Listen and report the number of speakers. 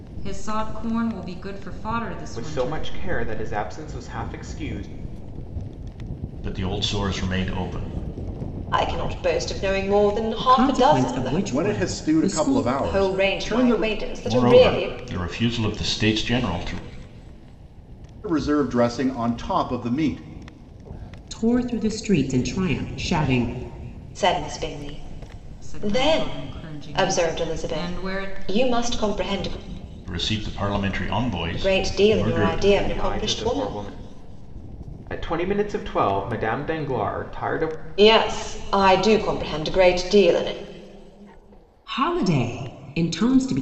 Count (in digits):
6